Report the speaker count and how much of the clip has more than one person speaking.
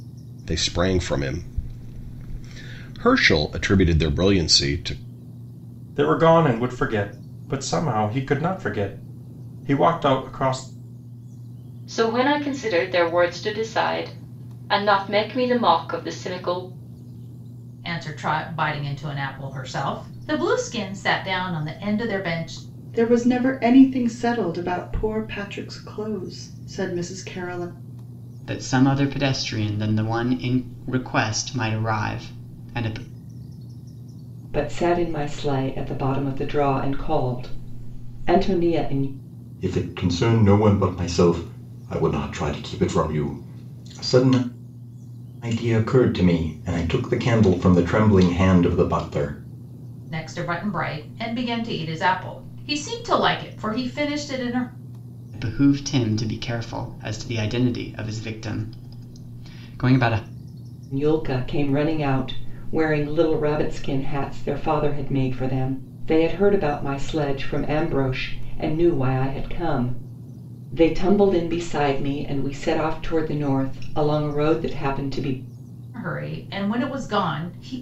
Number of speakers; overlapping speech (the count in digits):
8, no overlap